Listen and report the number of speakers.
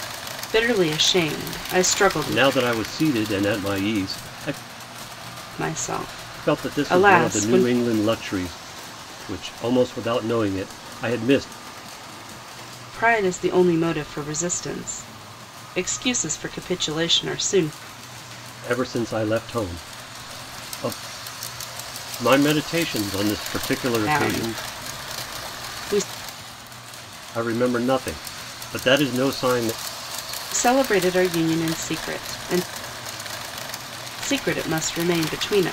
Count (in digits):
2